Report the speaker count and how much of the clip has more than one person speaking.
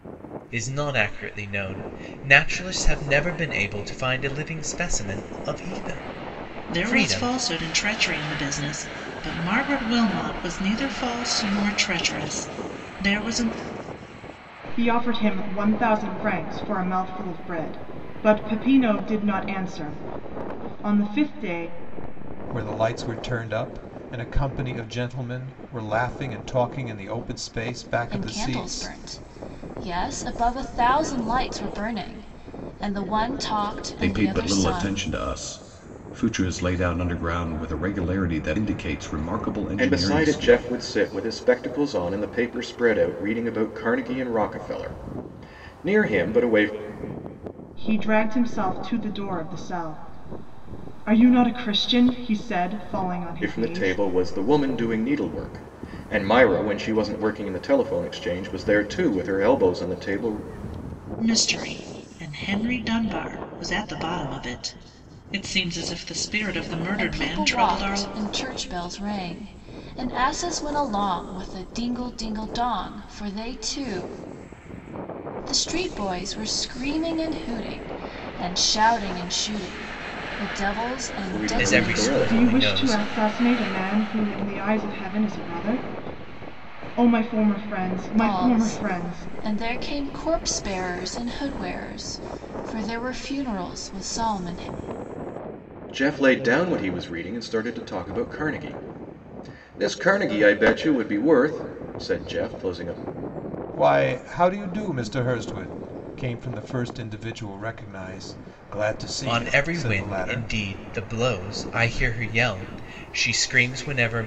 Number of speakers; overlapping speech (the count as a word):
seven, about 8%